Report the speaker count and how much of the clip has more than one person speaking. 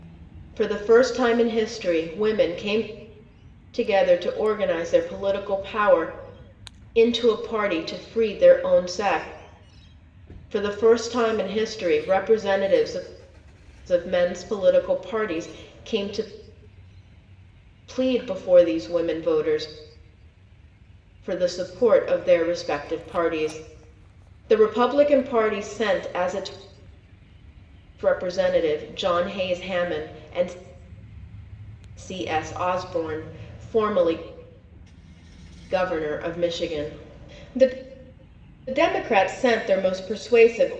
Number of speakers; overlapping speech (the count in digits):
1, no overlap